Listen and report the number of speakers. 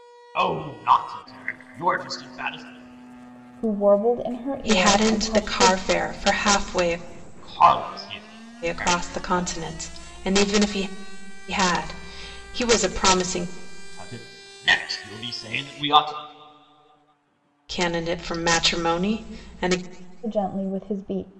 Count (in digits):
3